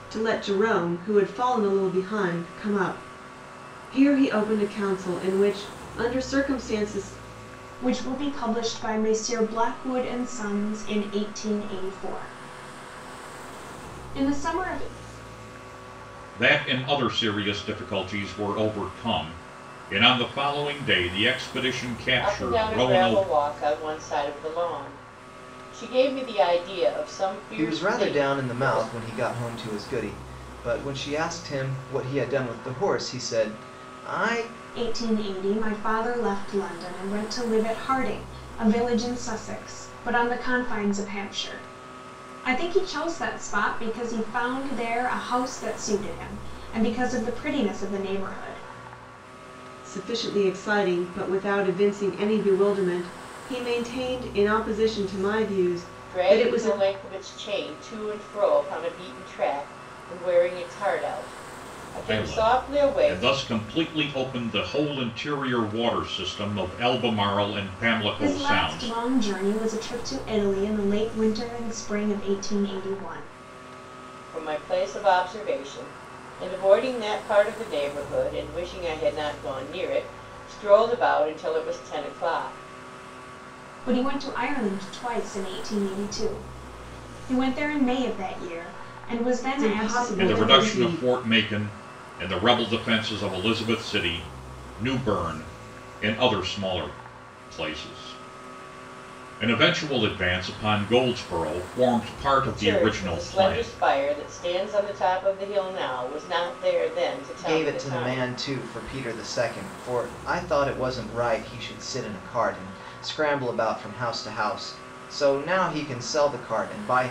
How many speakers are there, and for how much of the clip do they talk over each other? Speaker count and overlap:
5, about 8%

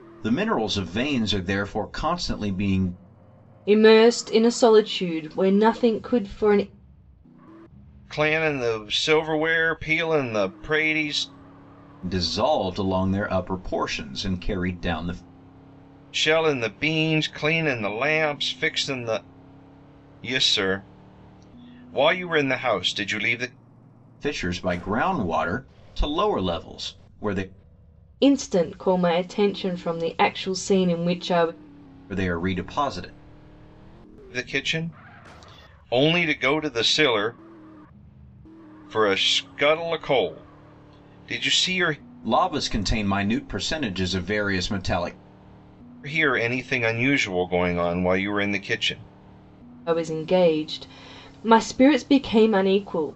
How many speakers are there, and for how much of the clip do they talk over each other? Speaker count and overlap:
3, no overlap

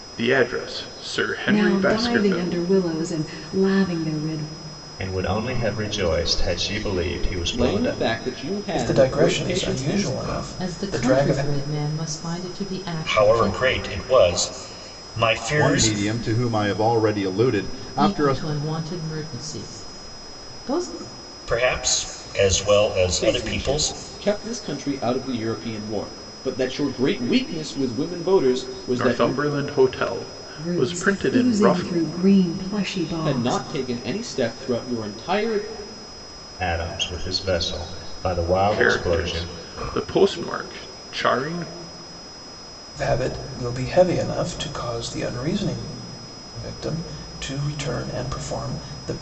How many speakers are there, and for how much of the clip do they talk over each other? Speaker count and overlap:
8, about 19%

